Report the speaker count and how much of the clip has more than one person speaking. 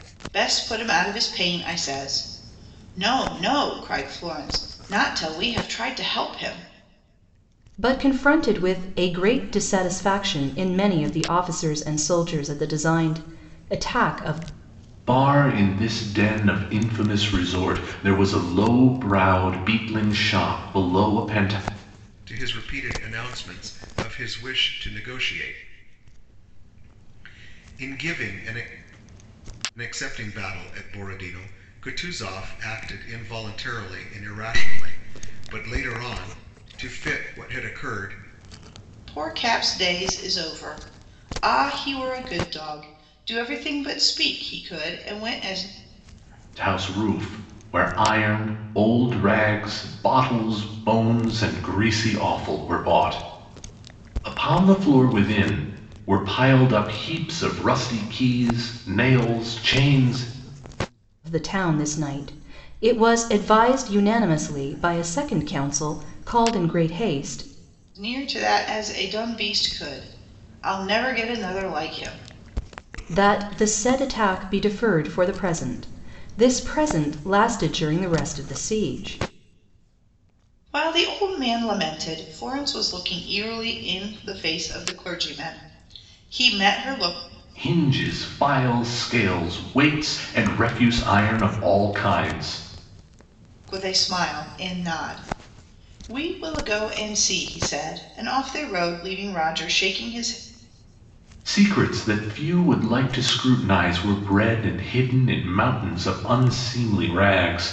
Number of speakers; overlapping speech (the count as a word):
four, no overlap